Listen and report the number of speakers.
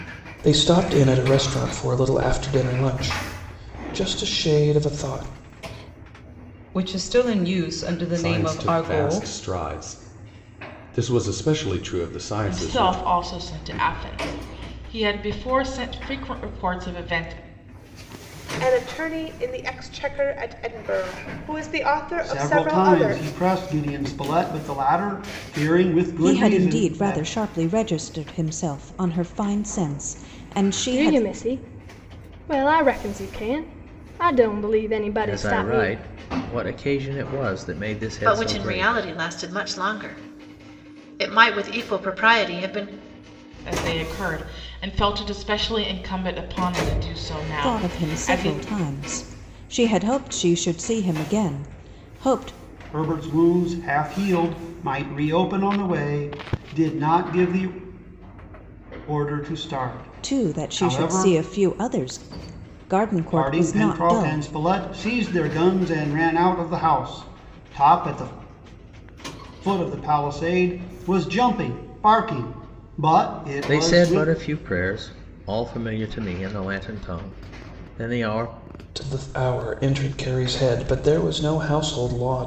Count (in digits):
10